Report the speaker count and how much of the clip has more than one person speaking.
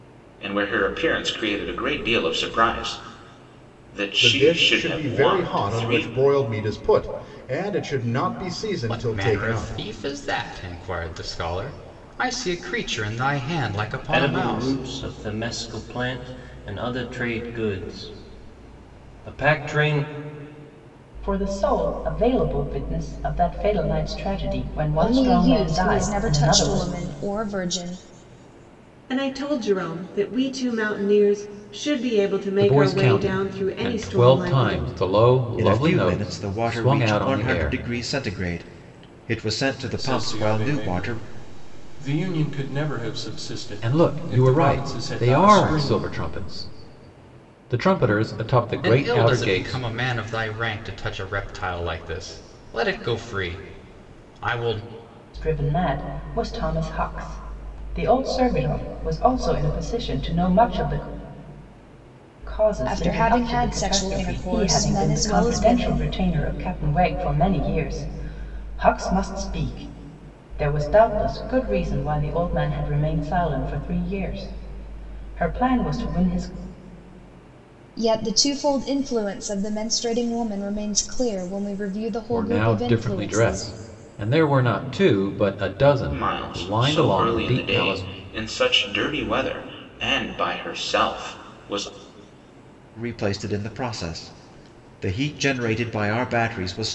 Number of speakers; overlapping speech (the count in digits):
10, about 22%